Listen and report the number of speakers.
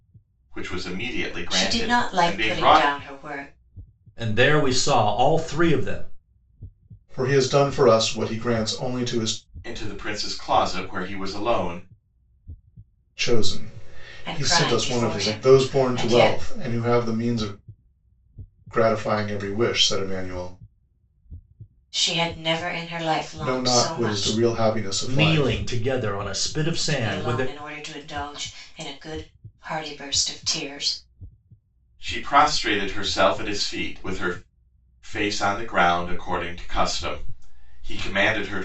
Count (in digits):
4